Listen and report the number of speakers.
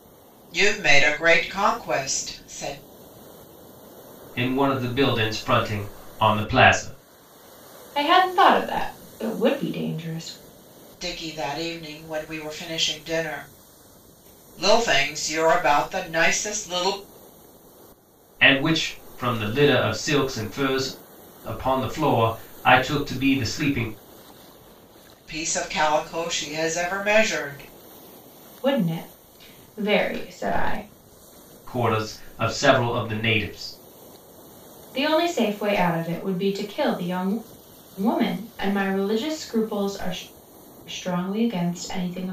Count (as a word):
three